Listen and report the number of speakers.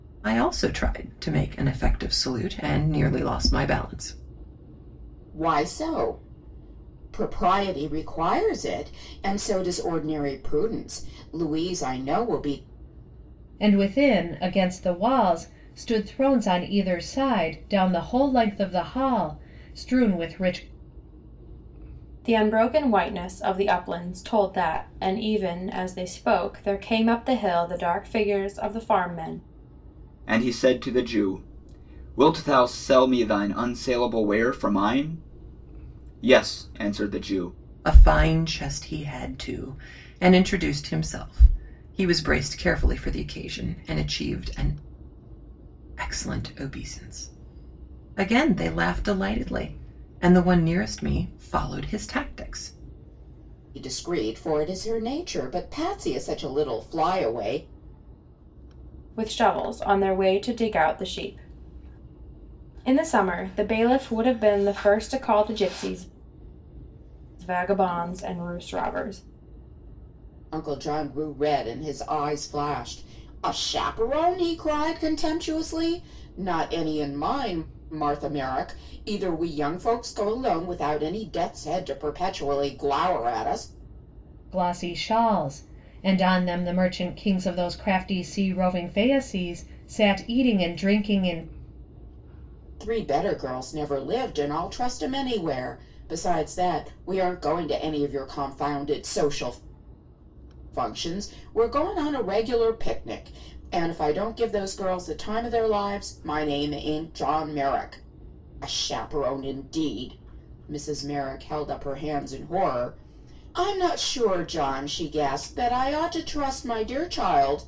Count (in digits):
5